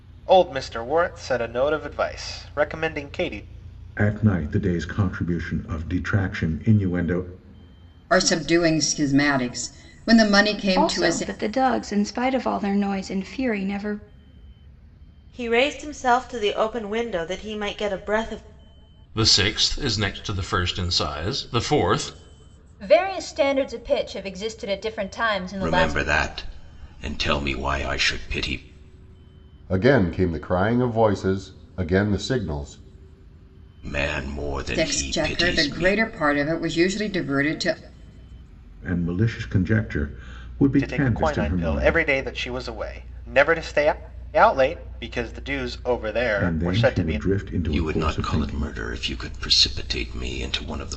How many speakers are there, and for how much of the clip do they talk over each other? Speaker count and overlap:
nine, about 11%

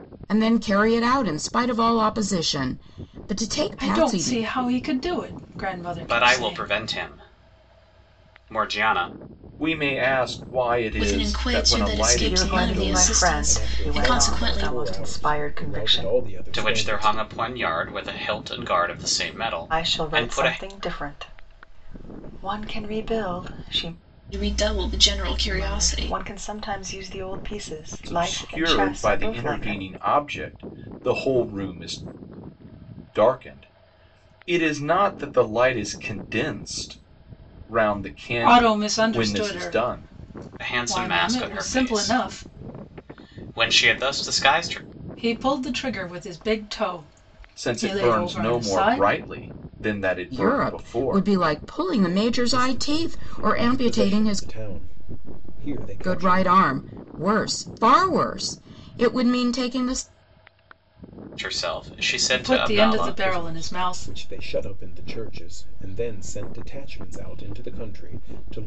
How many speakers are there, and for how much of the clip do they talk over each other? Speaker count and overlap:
seven, about 31%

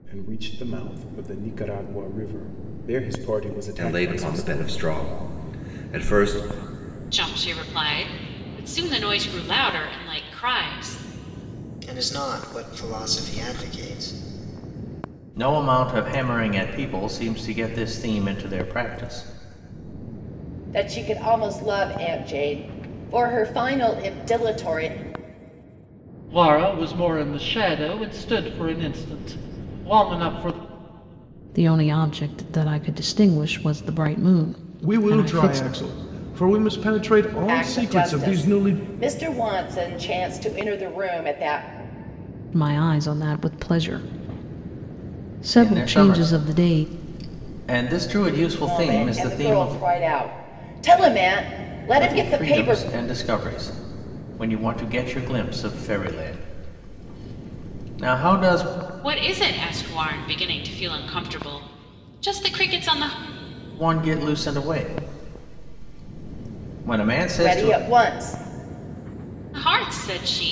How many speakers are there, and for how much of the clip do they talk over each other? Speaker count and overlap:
nine, about 10%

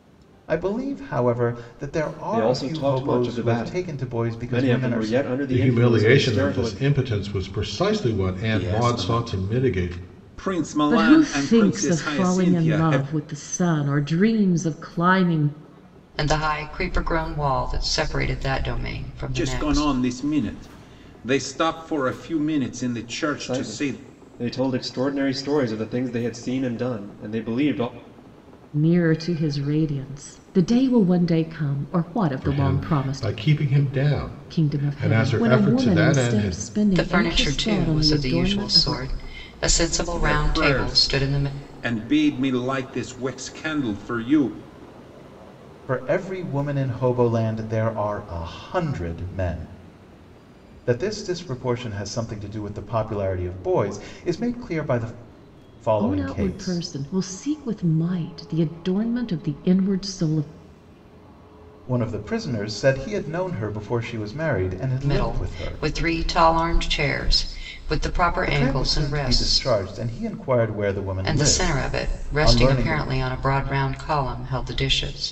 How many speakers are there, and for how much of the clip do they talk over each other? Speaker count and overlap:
six, about 28%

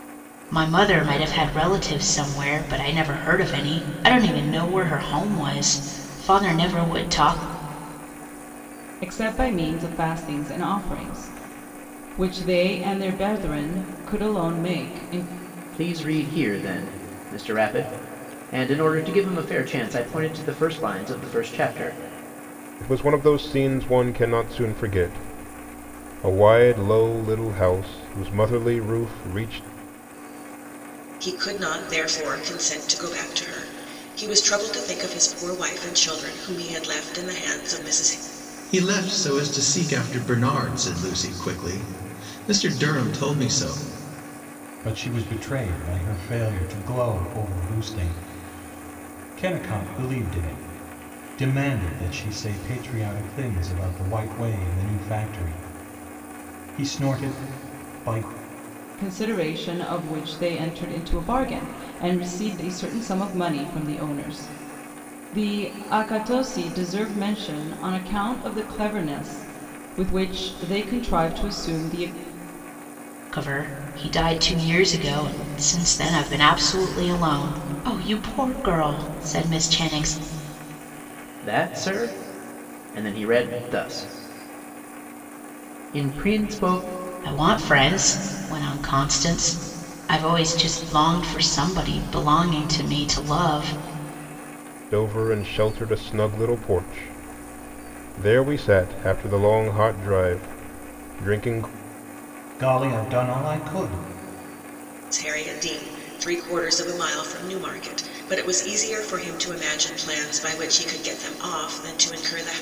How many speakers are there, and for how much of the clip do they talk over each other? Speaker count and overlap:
seven, no overlap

